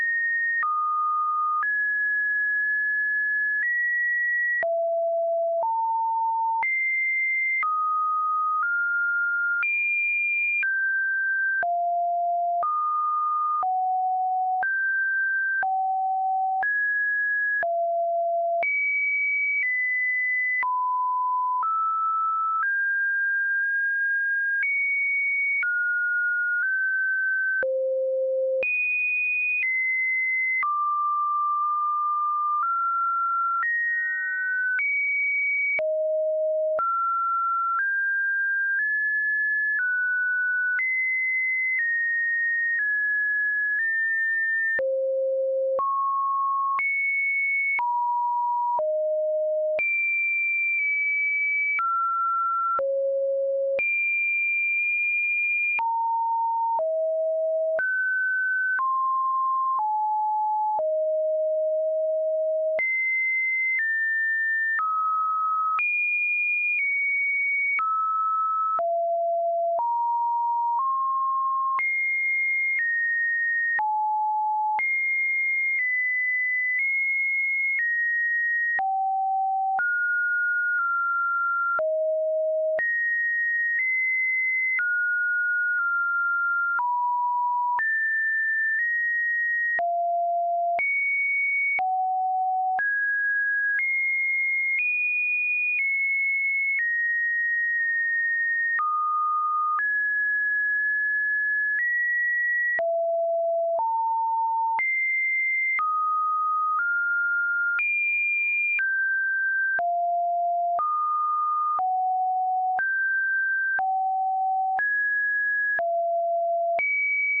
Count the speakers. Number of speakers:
zero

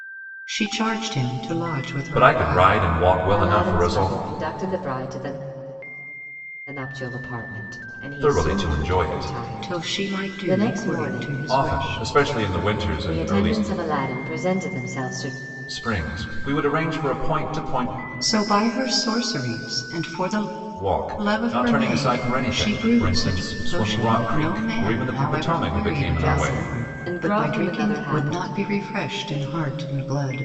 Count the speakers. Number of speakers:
three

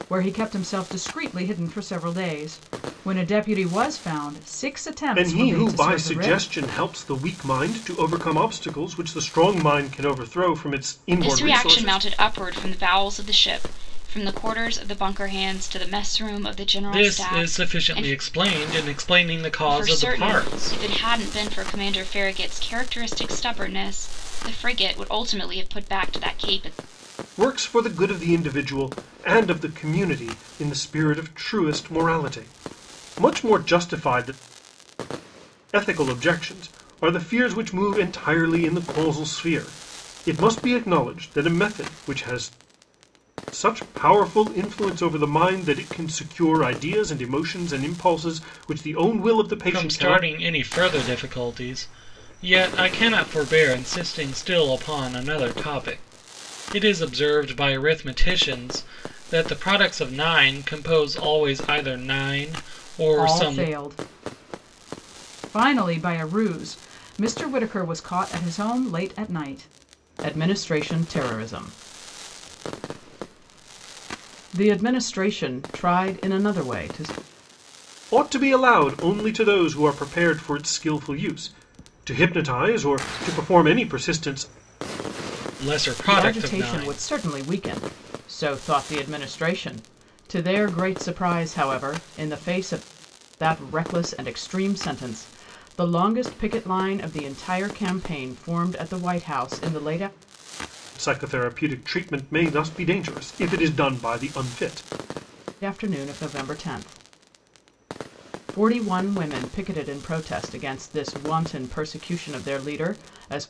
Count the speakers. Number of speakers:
four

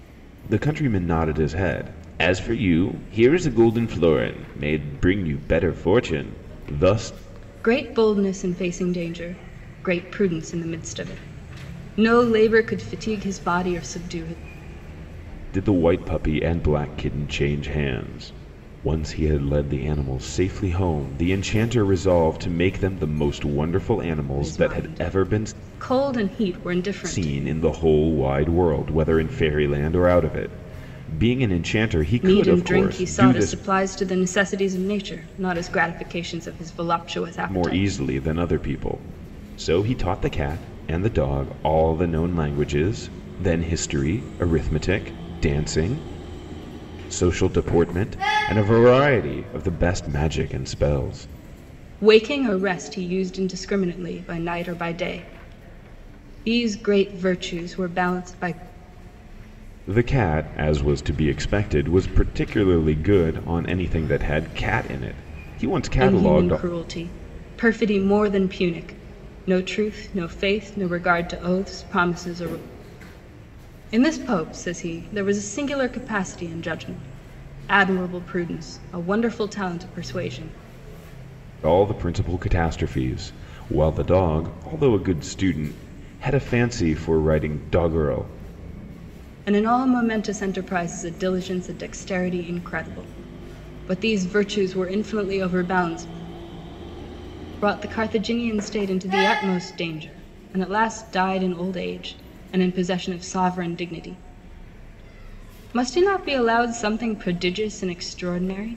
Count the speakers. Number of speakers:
two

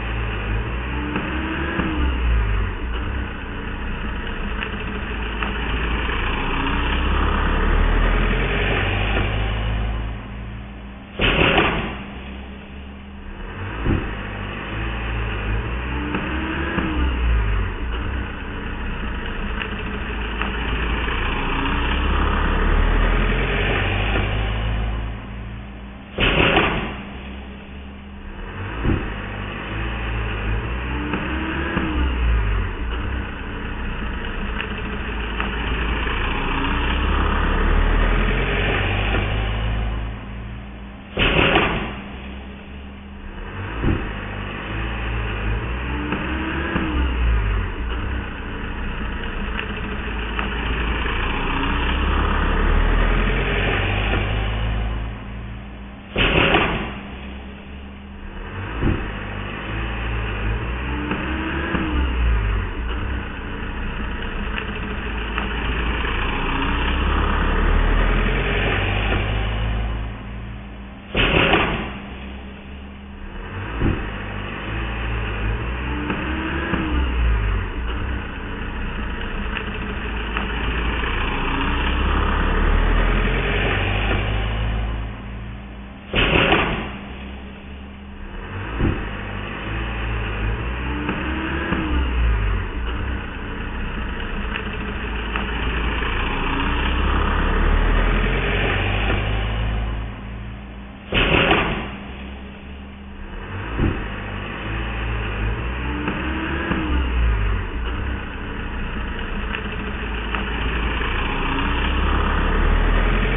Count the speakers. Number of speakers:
zero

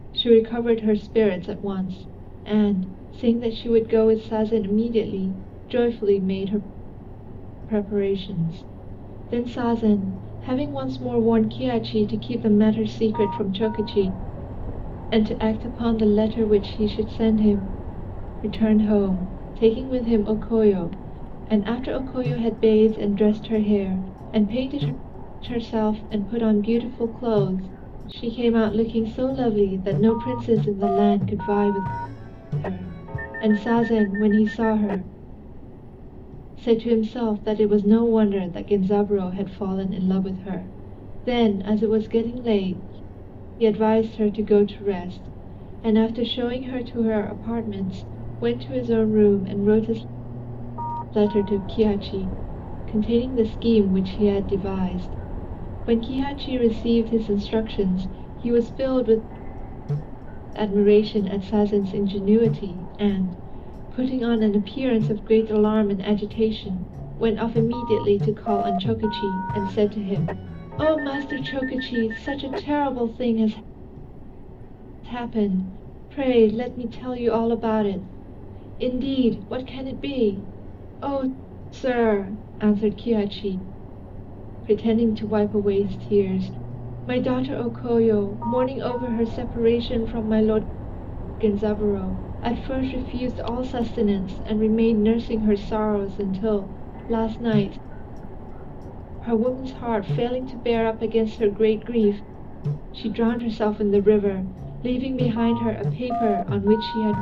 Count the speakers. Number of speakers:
one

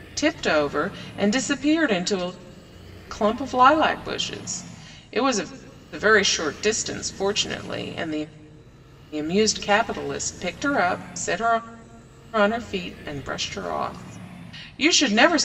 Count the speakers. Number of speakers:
one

